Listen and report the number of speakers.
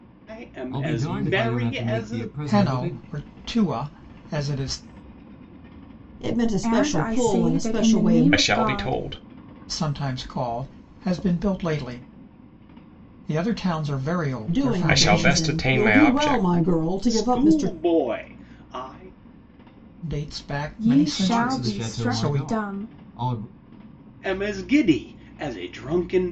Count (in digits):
6